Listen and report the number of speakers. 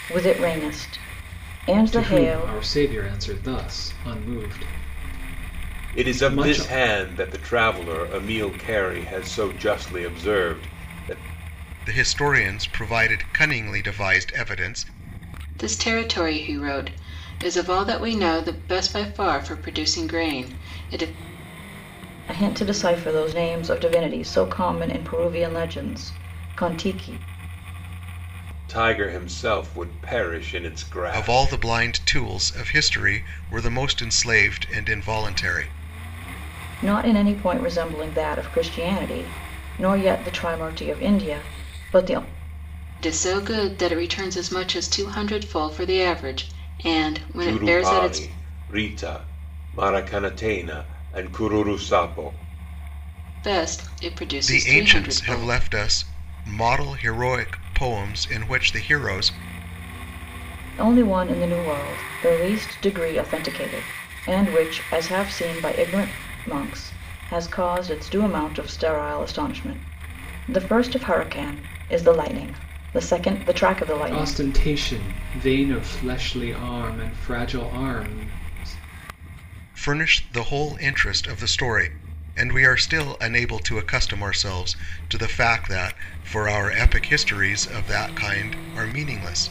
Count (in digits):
5